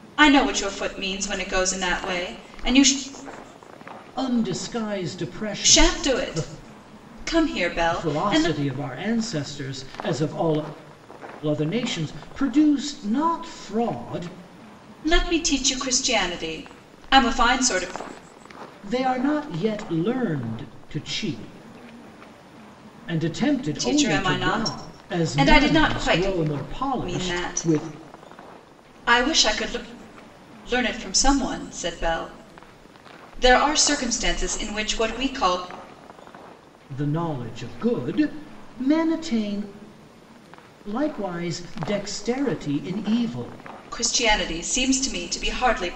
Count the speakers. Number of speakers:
two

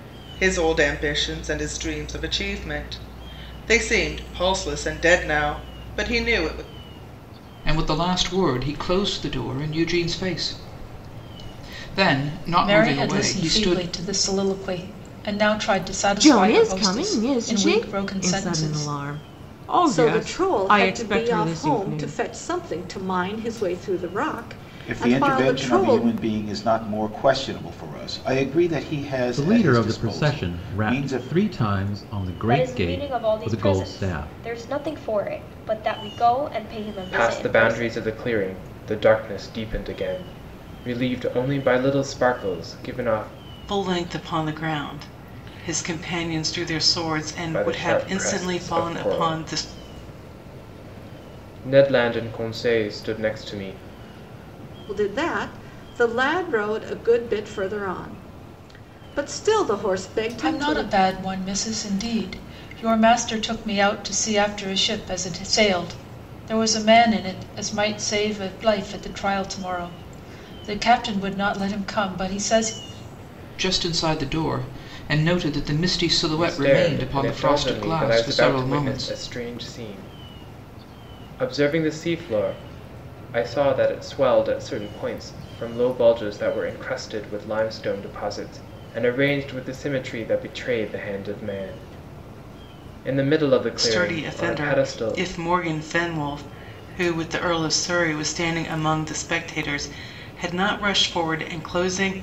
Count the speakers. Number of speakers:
ten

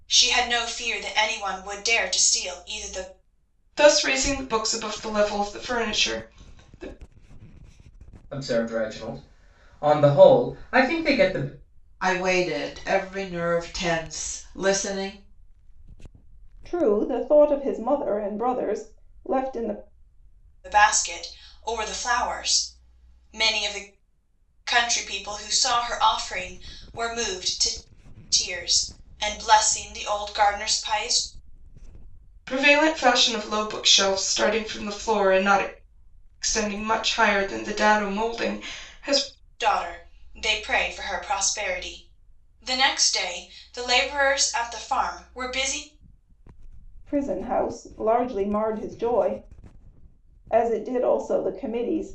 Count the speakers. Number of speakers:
five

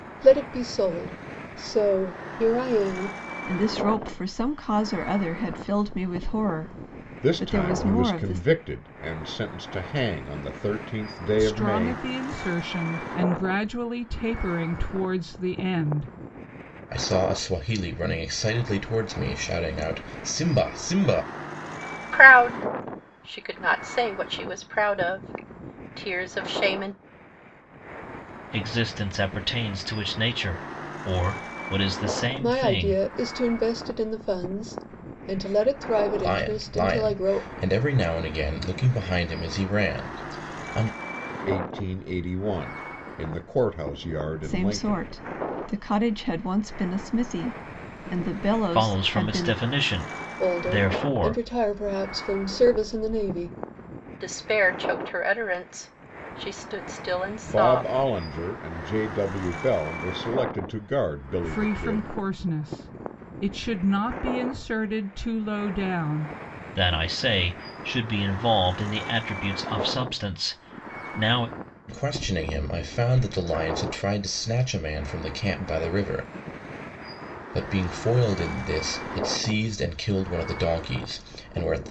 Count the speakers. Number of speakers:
seven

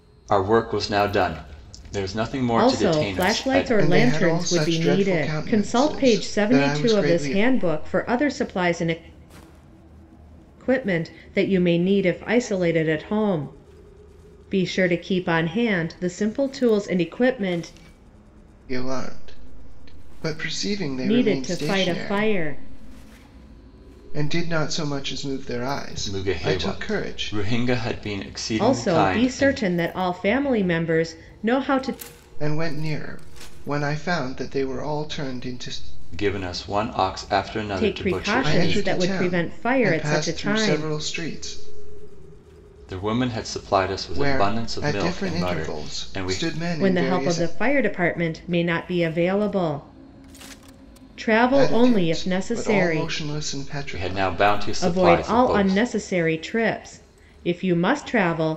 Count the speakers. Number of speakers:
three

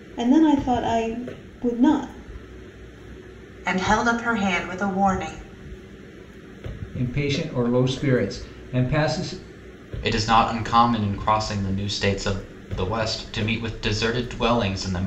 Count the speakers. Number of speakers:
four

